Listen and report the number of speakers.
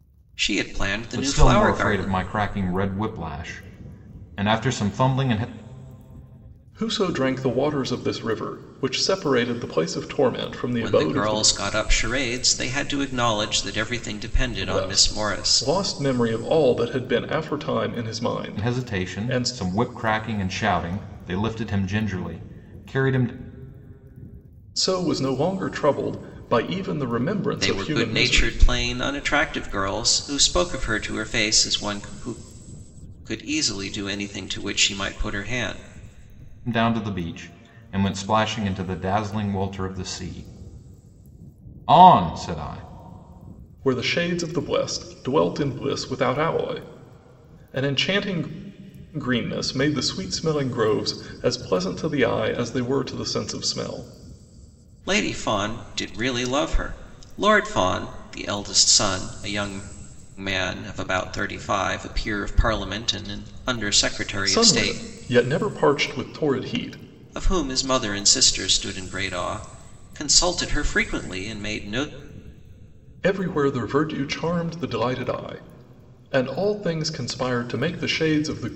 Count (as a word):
three